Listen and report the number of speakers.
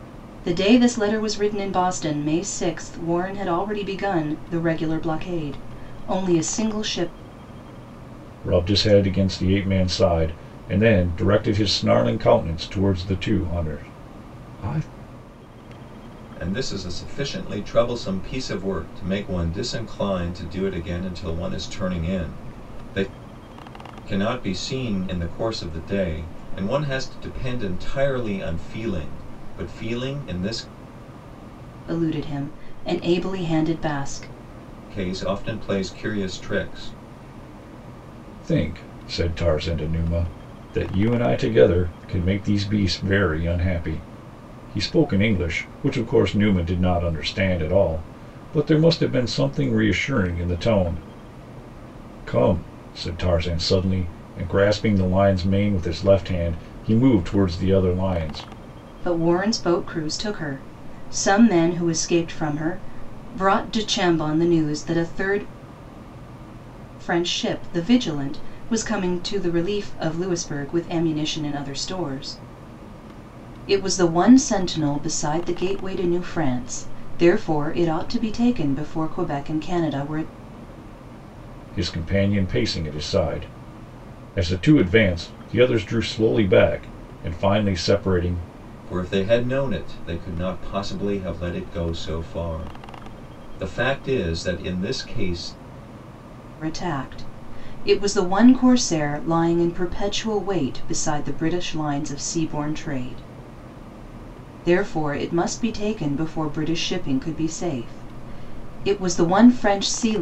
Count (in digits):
3